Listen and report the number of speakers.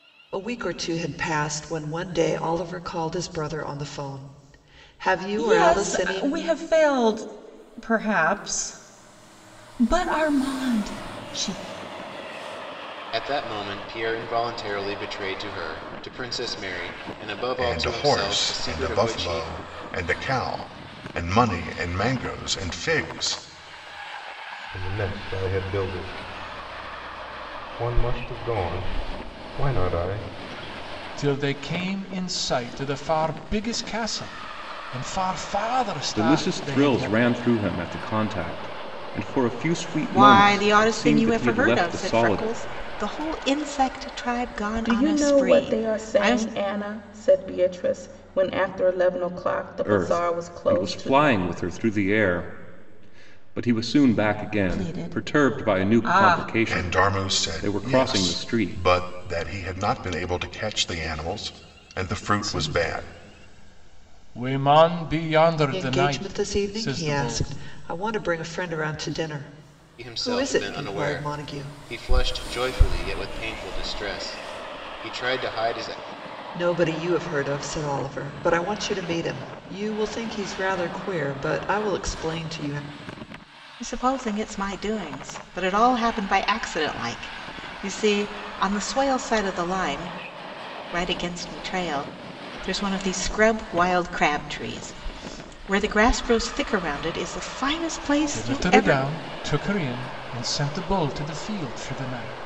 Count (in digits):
9